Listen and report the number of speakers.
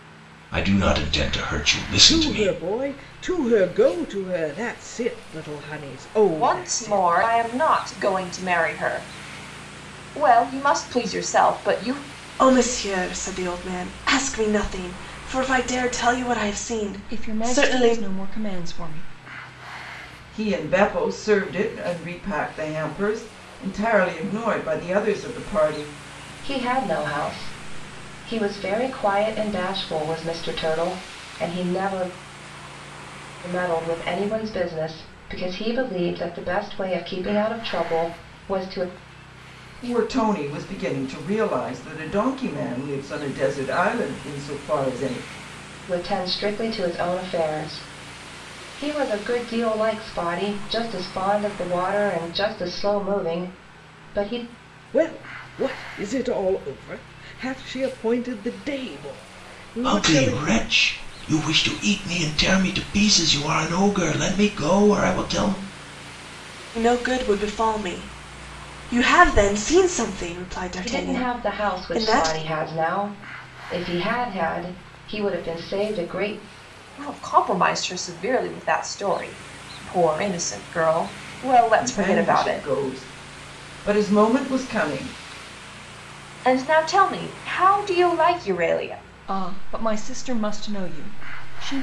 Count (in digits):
7